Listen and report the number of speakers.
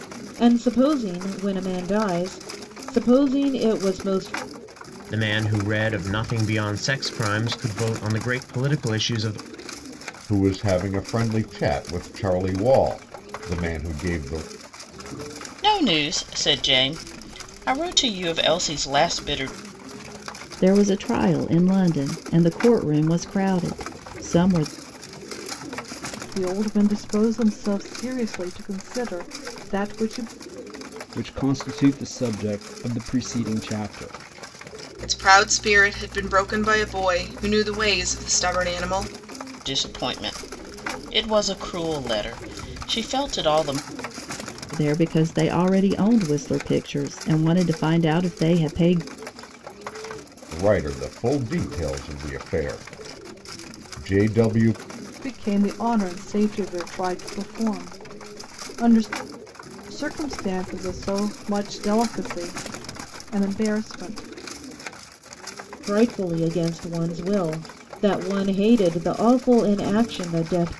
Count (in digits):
8